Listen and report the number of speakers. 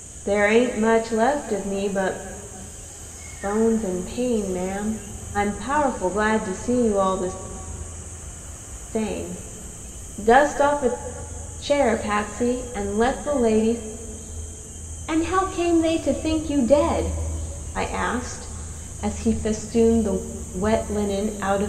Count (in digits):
1